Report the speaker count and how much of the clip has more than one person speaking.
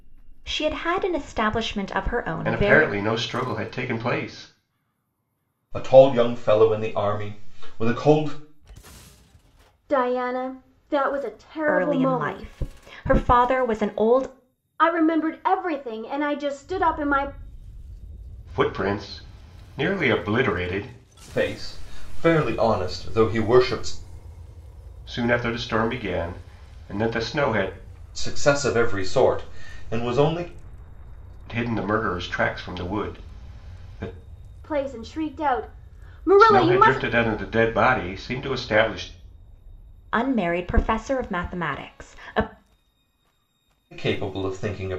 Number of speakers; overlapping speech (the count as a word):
four, about 5%